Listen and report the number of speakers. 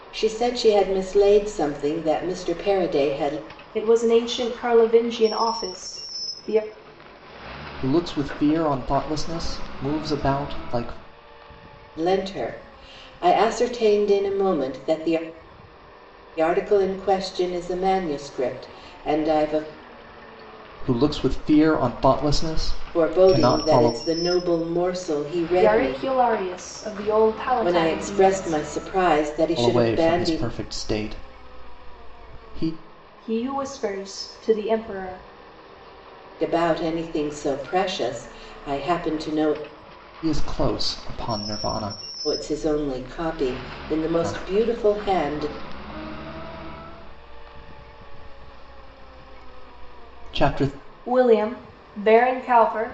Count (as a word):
three